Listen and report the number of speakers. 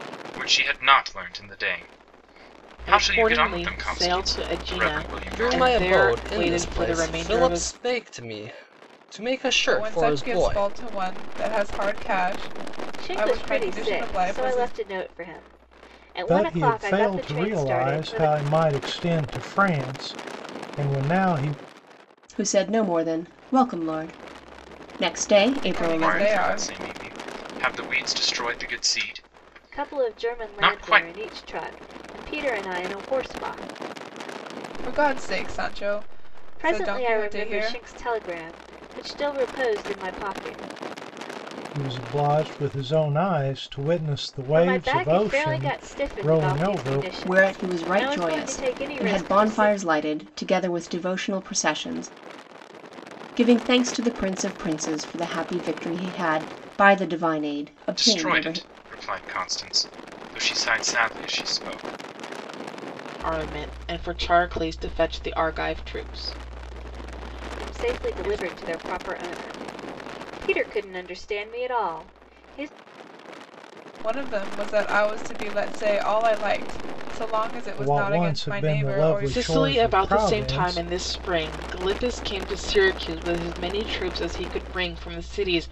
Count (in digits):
7